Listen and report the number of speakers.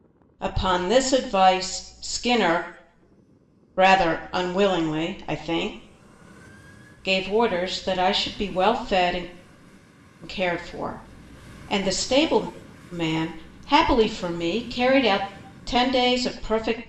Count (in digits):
1